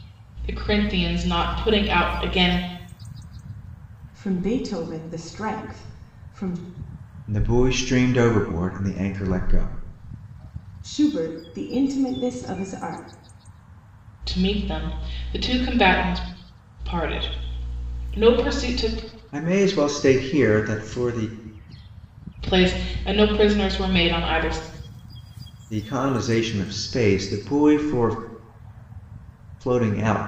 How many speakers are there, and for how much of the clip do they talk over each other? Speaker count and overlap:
3, no overlap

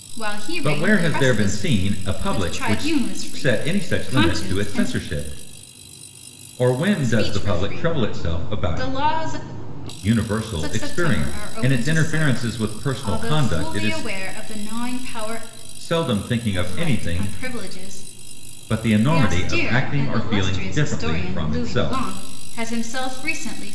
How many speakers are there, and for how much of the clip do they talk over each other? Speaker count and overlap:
2, about 53%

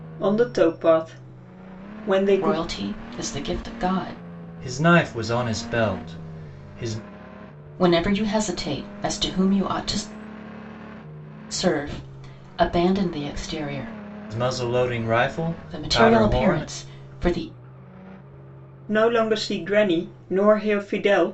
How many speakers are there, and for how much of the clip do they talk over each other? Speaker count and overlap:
3, about 6%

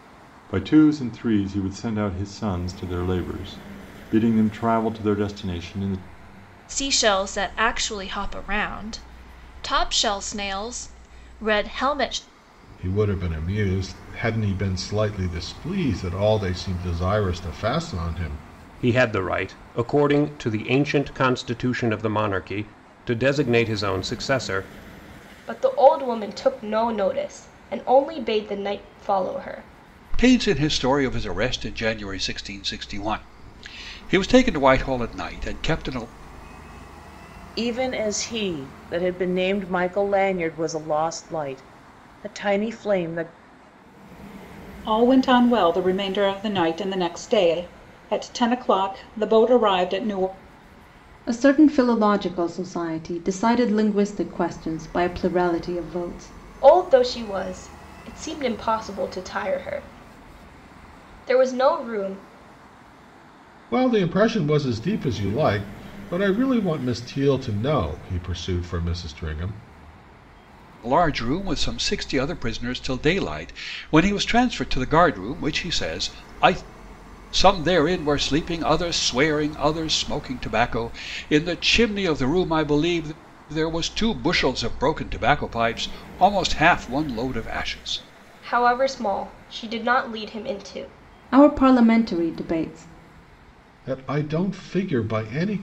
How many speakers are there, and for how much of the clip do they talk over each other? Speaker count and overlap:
9, no overlap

